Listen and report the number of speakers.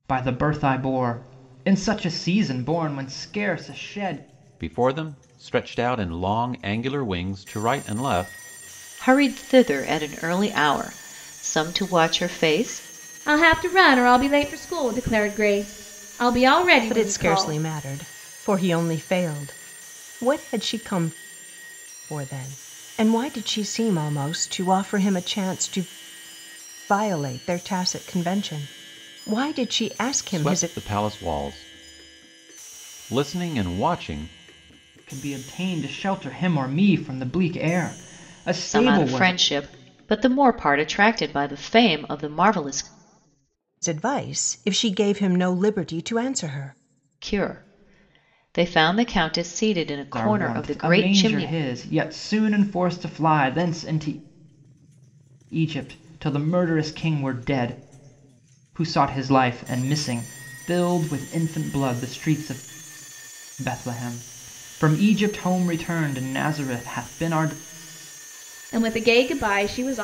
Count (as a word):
five